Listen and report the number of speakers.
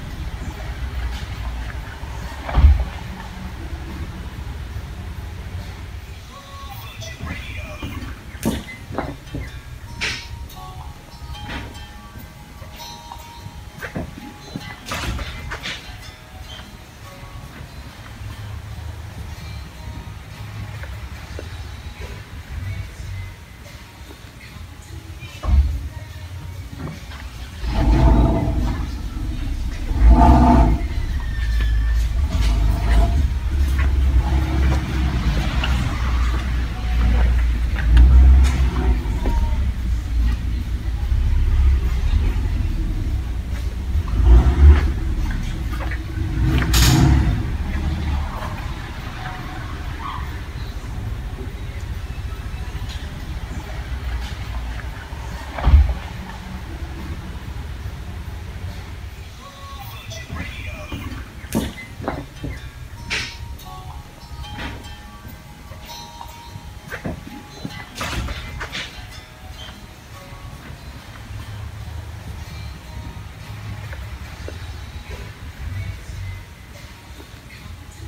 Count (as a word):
zero